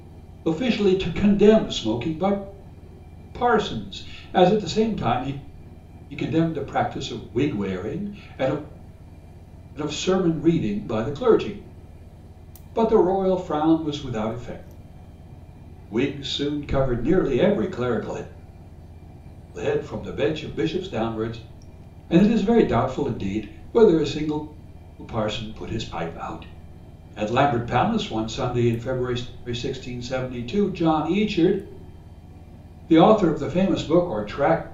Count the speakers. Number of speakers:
1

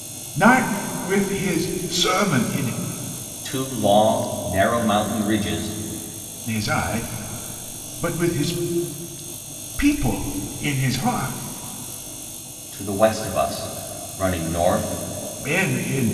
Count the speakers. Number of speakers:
2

